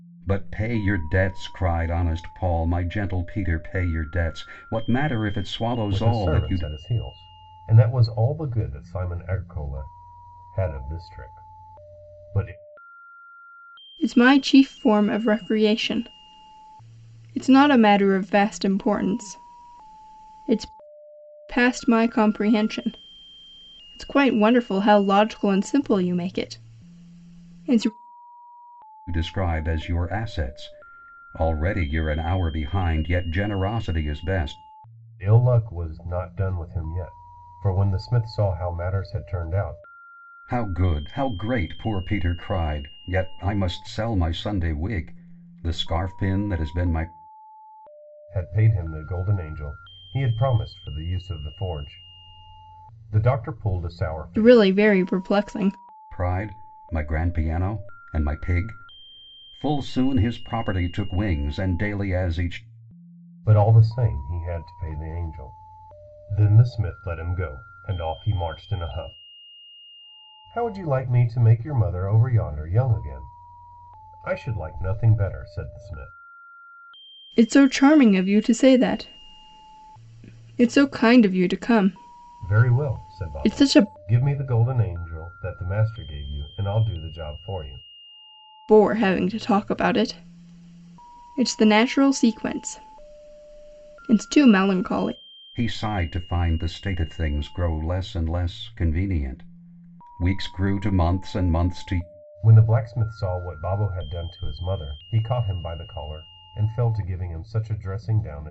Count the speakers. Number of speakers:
3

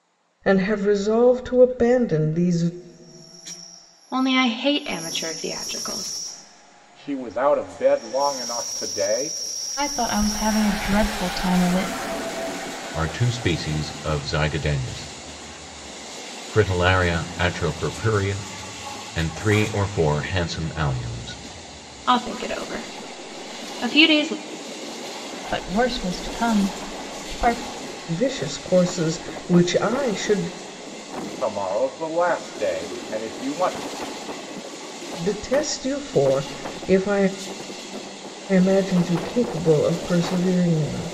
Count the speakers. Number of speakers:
5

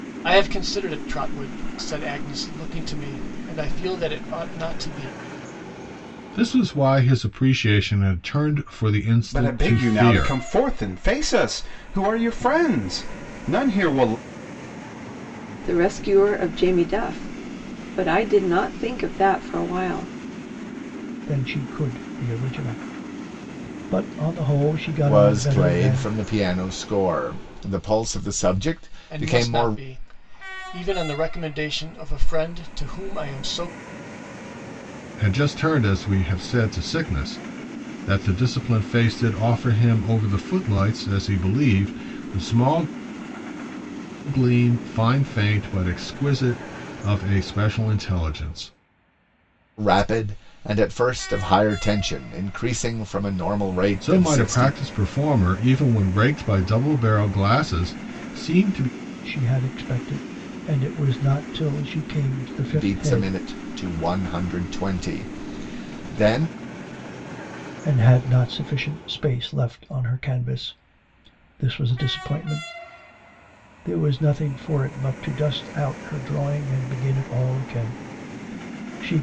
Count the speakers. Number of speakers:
6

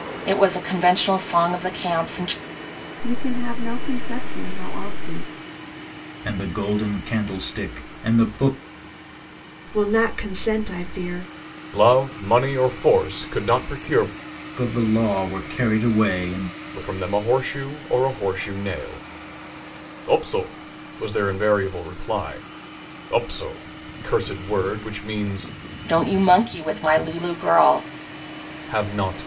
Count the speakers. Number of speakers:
5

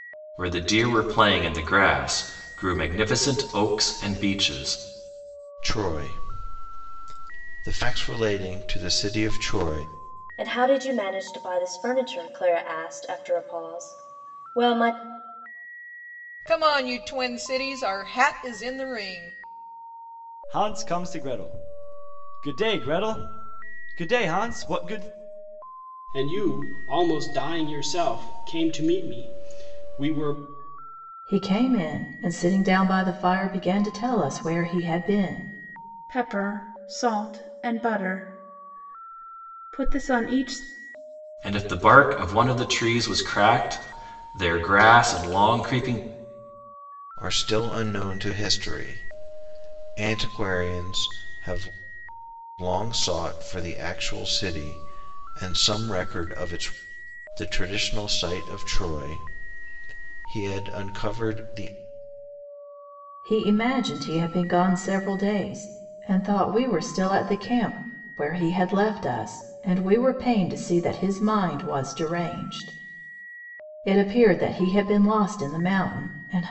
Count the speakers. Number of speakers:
8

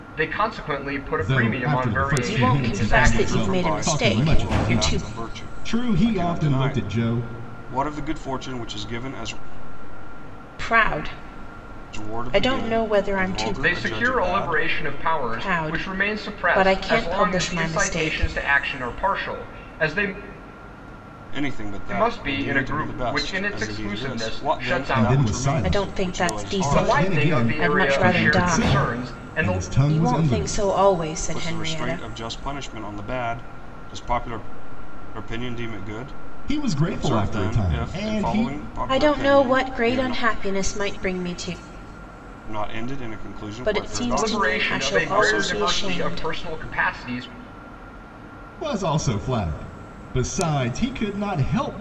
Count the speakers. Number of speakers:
4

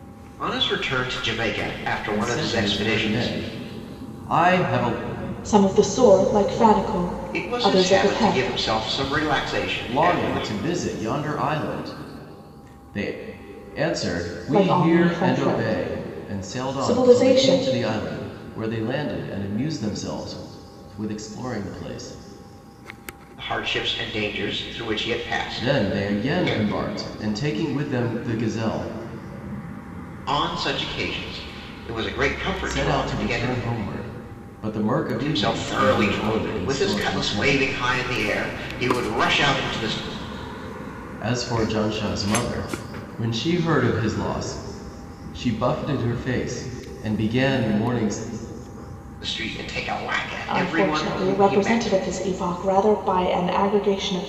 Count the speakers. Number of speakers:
3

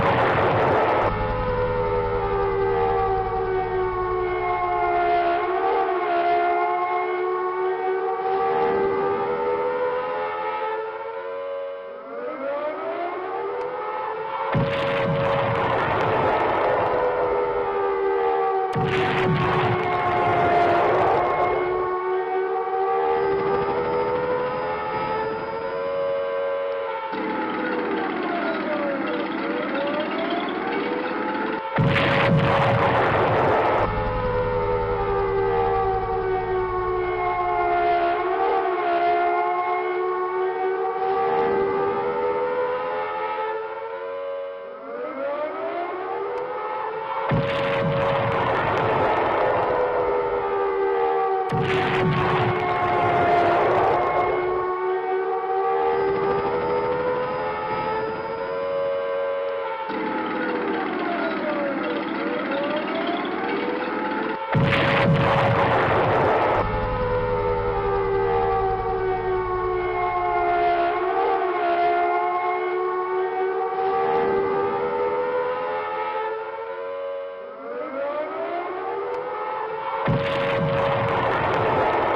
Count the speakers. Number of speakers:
0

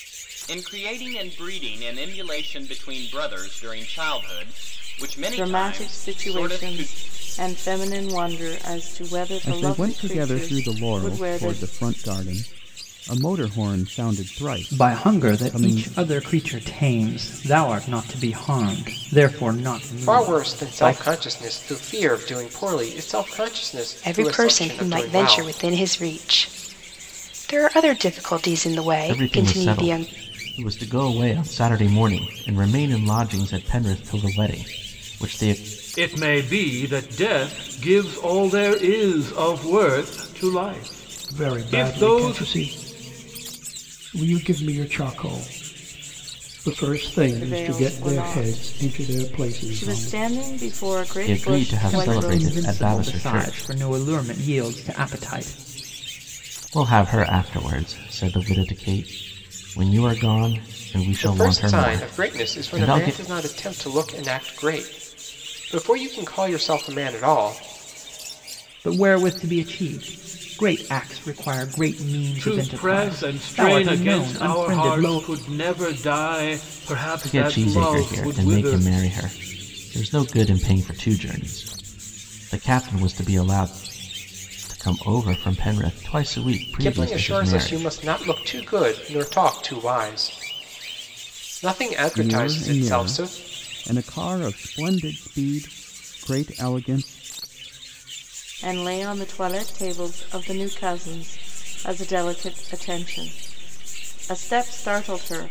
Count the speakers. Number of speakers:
9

